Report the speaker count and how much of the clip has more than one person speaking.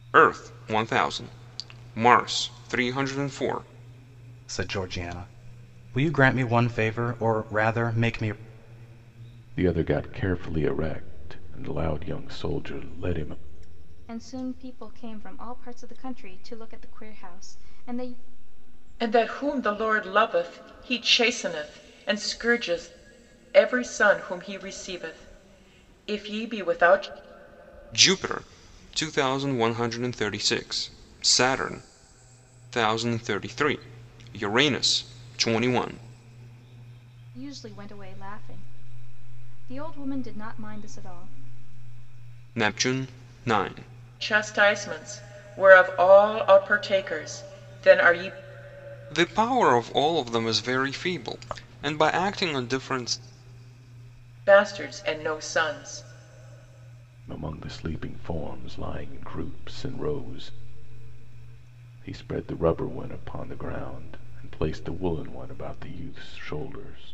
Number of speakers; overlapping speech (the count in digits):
5, no overlap